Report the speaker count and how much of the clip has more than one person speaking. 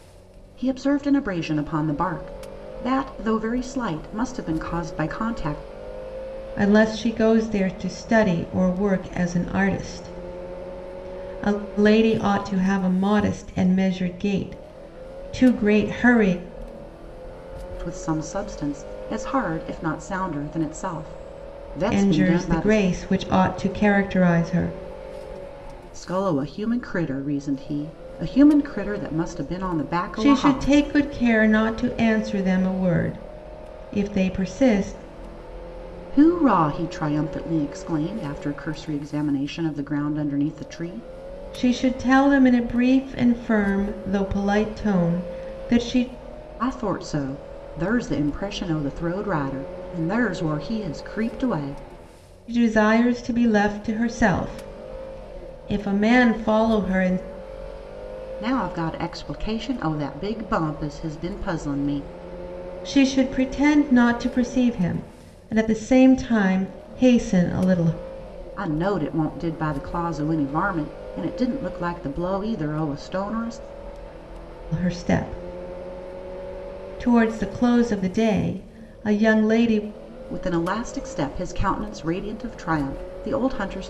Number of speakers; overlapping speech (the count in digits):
2, about 2%